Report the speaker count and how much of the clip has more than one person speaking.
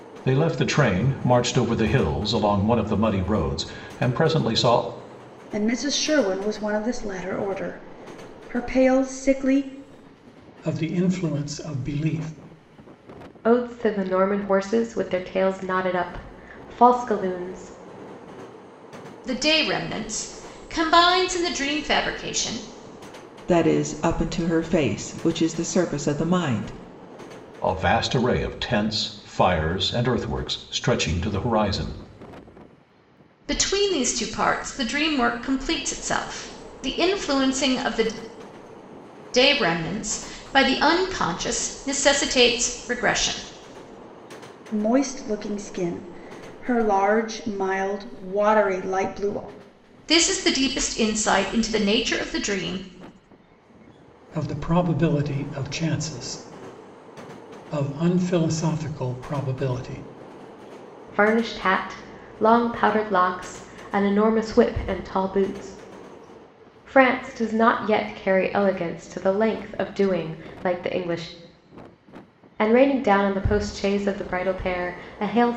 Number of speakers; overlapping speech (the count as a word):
six, no overlap